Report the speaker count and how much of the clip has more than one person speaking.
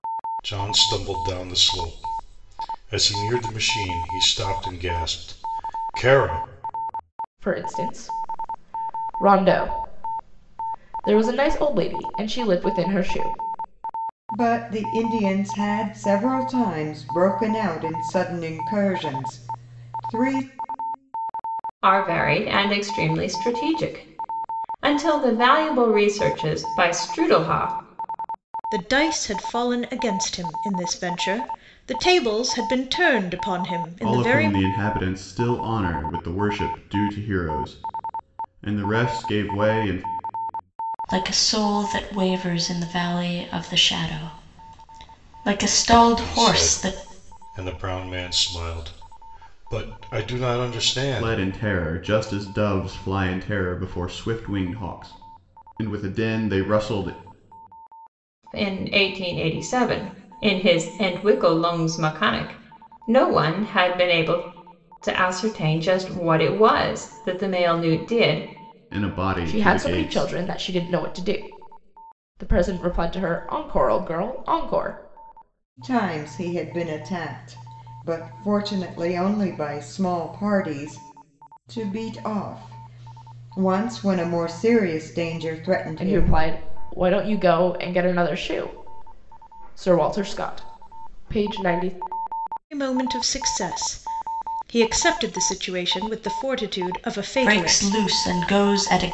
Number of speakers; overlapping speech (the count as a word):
seven, about 4%